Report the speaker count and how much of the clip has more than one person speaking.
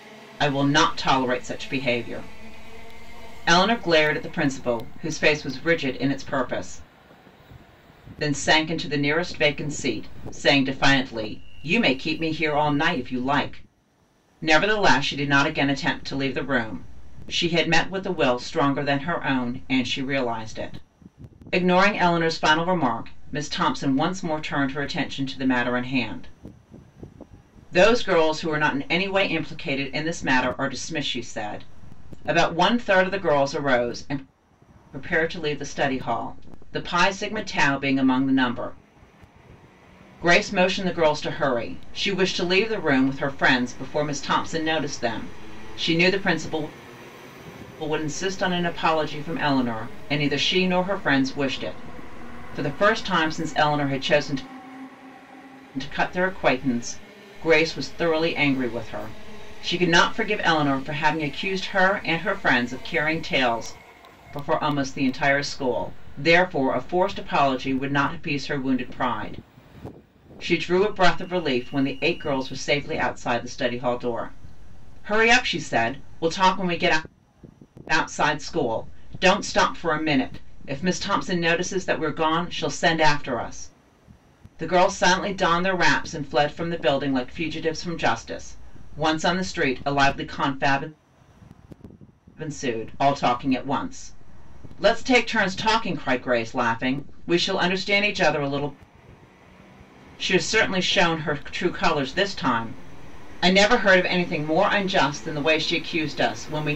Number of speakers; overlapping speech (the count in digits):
1, no overlap